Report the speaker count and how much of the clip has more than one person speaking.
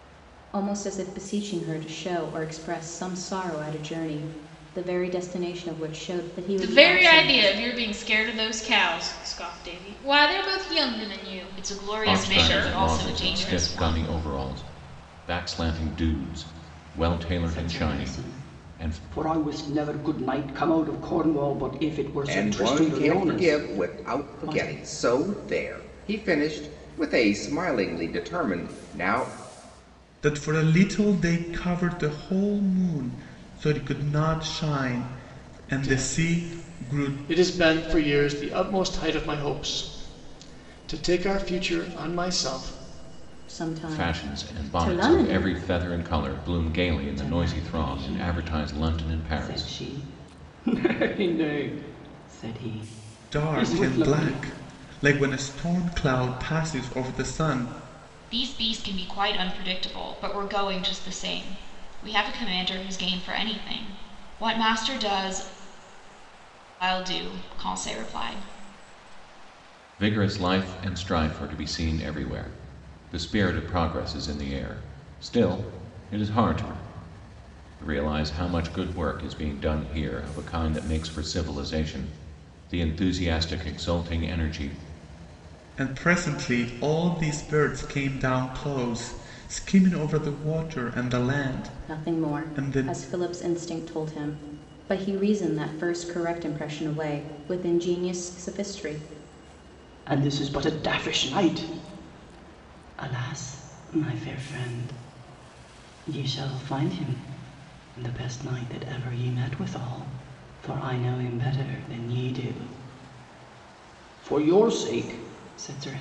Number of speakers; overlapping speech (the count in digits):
8, about 13%